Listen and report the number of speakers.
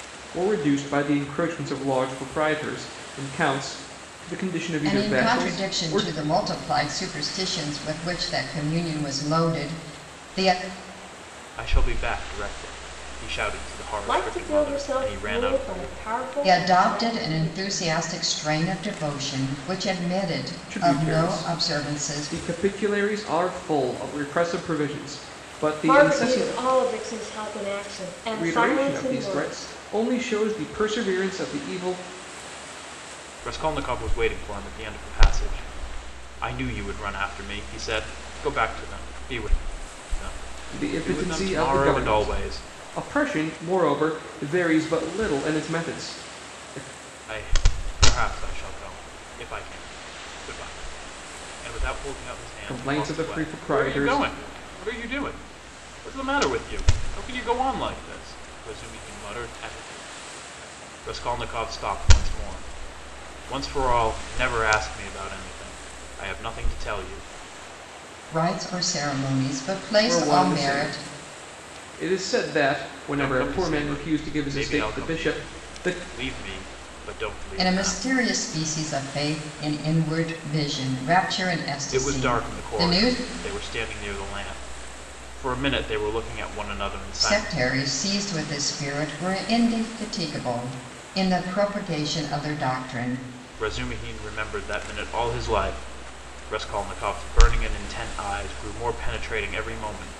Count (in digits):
4